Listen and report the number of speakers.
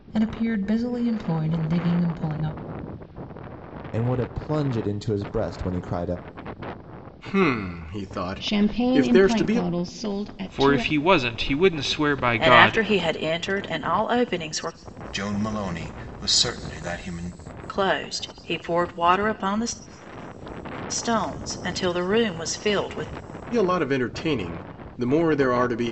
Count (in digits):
7